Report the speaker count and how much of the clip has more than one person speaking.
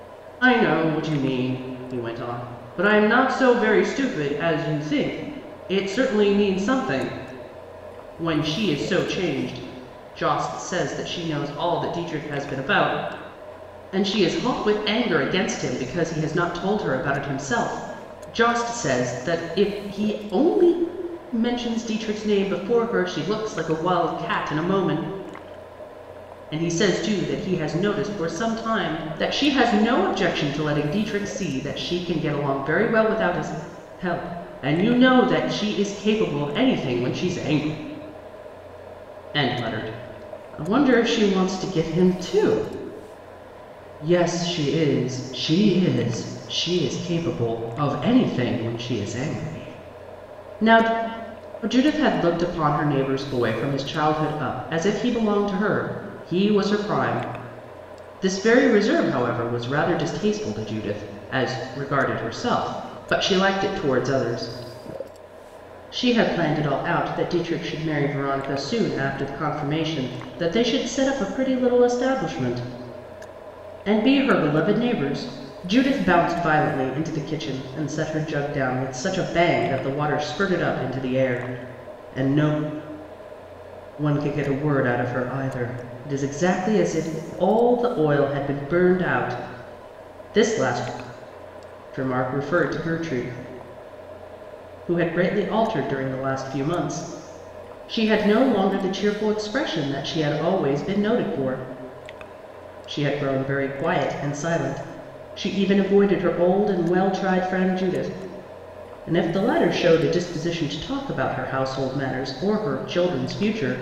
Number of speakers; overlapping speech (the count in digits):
1, no overlap